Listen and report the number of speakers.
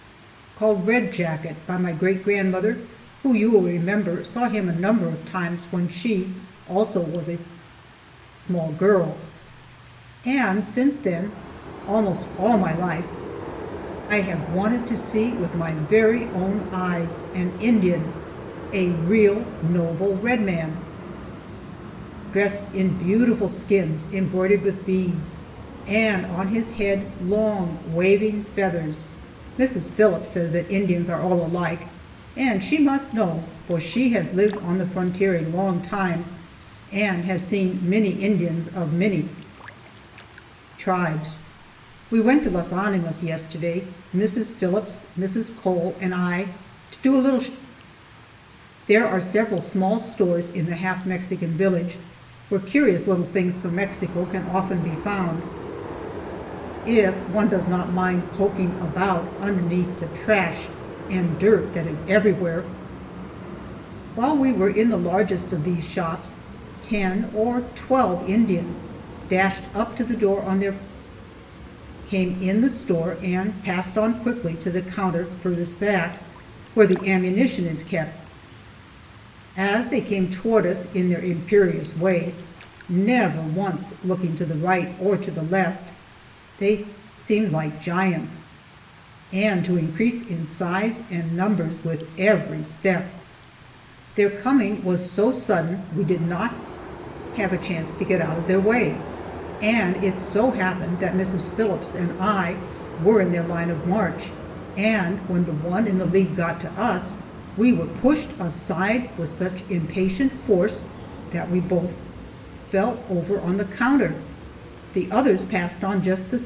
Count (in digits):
1